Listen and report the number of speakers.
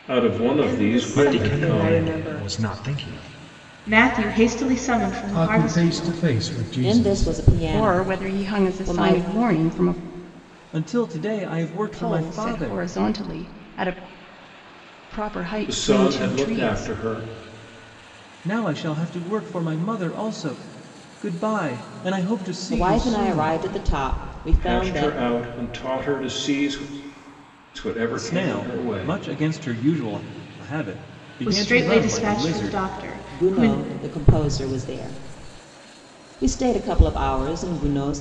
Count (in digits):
8